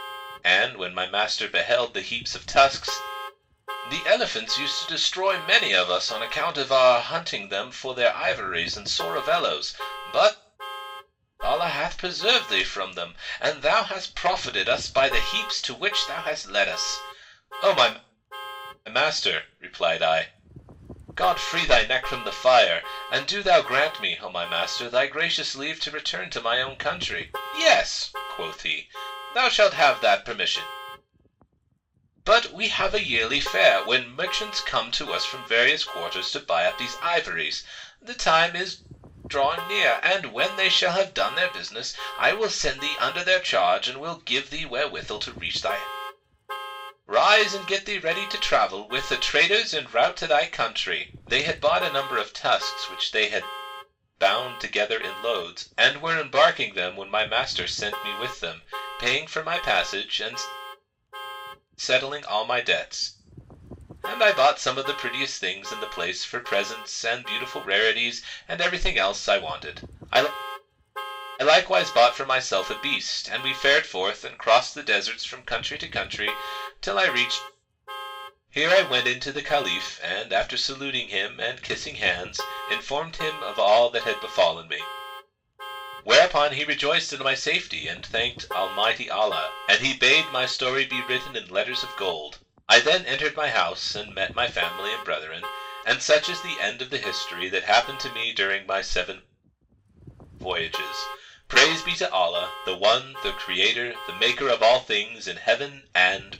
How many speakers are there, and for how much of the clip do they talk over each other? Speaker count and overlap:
one, no overlap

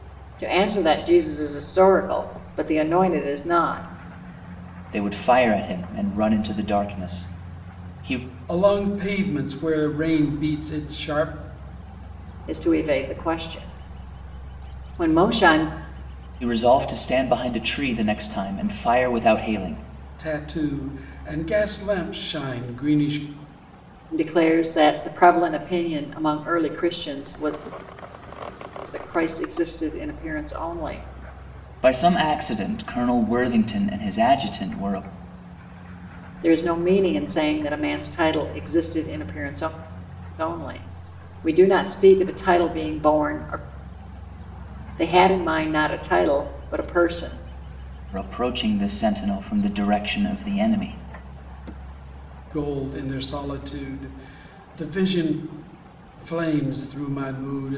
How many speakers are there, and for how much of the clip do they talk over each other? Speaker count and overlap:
three, no overlap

